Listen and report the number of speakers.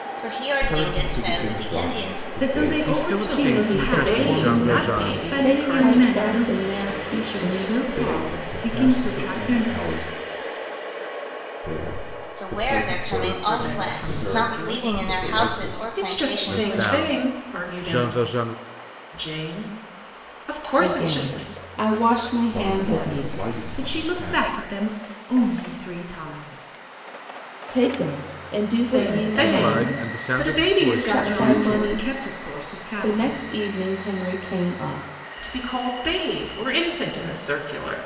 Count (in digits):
6